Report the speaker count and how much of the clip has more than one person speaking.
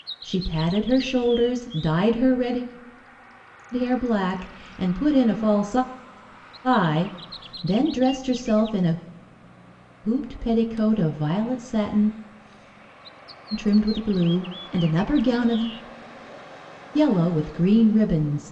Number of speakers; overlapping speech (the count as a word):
one, no overlap